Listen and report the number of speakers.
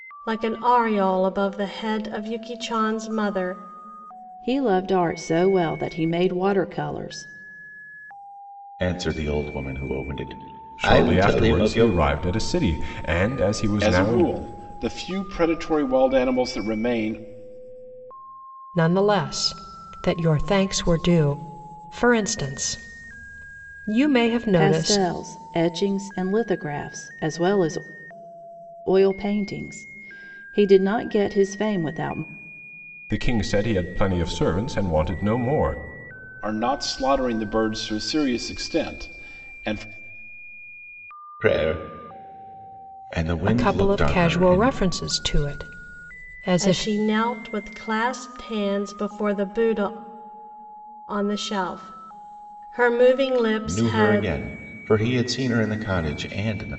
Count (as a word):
six